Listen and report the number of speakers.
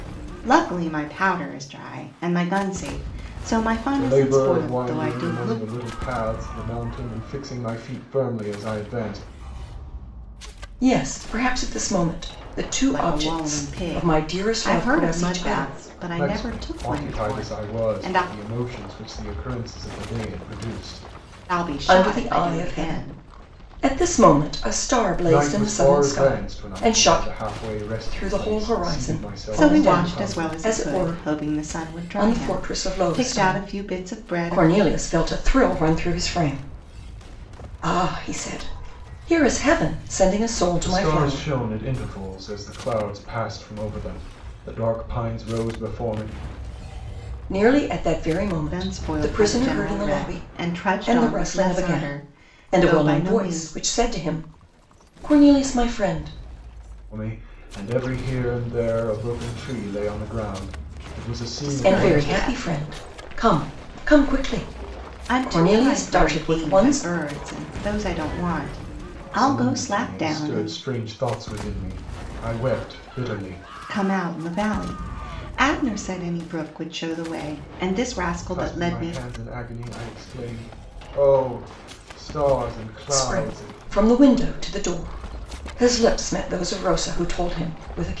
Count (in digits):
3